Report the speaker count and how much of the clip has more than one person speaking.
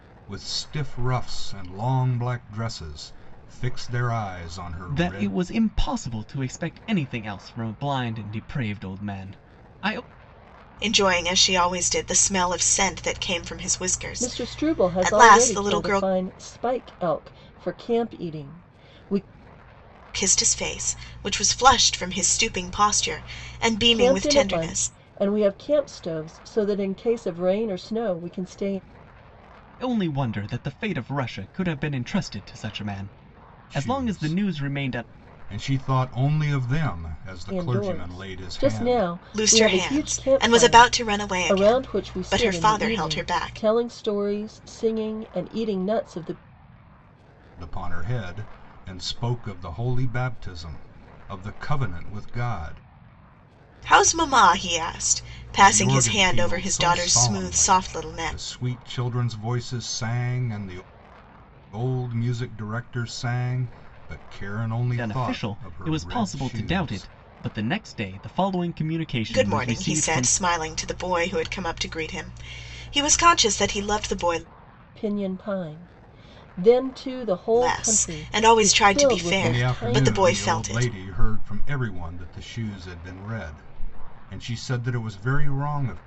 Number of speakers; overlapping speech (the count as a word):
four, about 23%